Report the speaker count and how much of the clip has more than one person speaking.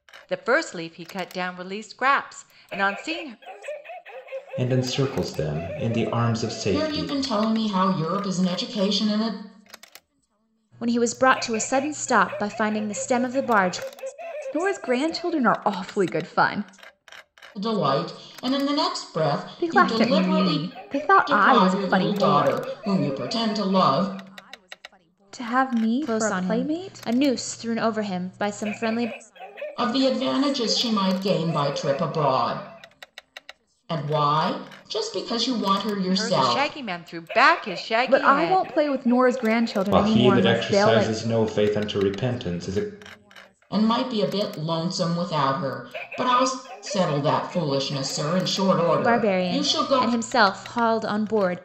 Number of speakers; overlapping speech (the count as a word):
five, about 15%